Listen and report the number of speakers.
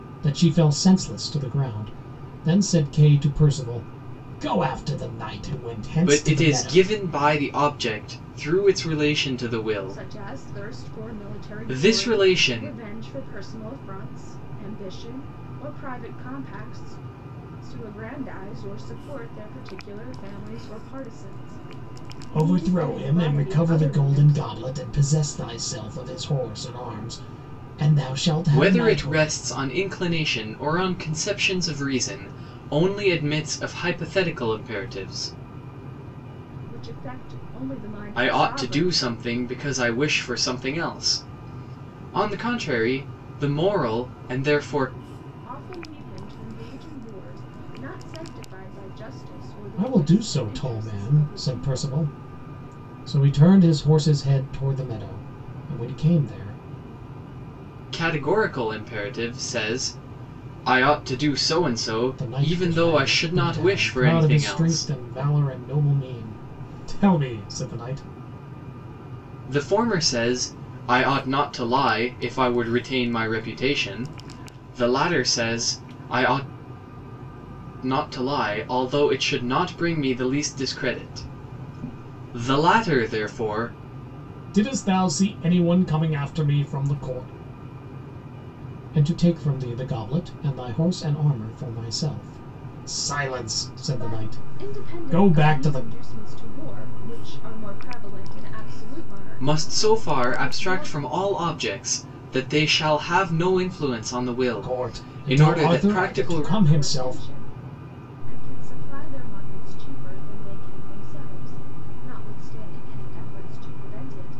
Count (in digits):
3